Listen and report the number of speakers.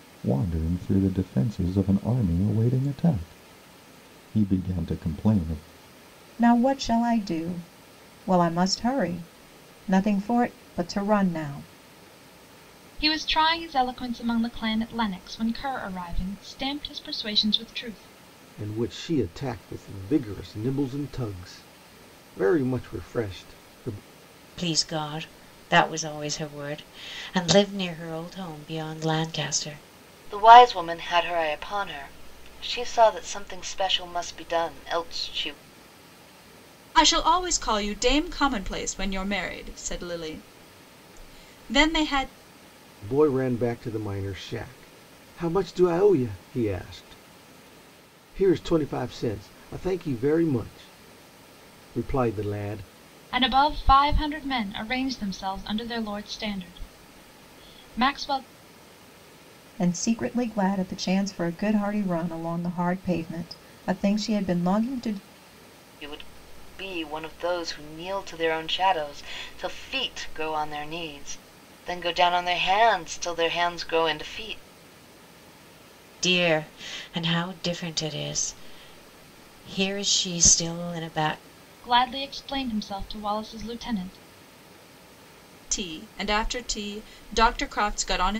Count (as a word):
seven